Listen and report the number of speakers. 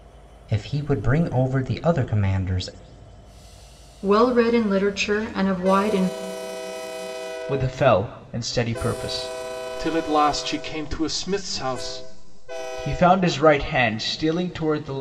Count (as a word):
four